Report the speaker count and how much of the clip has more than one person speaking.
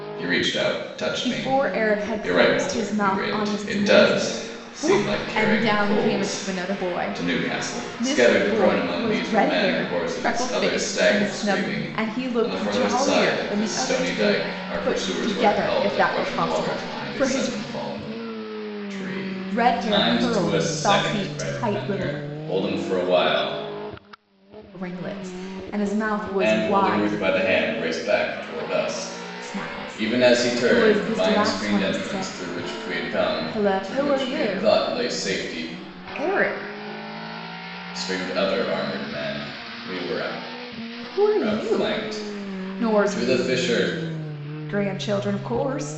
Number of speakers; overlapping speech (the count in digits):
2, about 58%